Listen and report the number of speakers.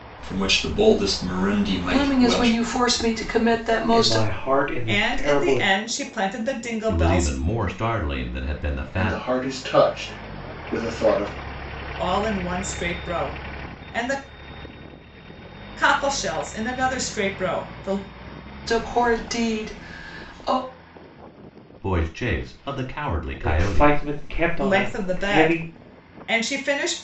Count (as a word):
six